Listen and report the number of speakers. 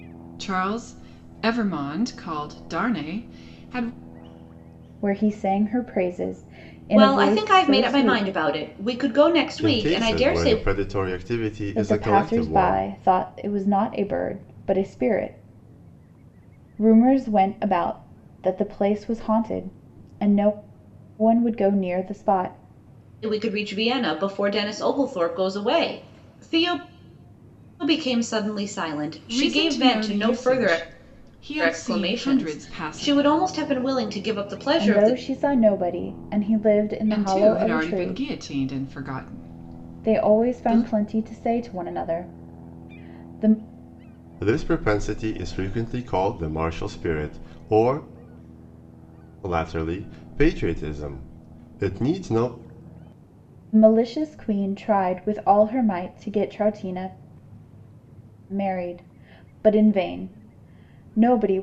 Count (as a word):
four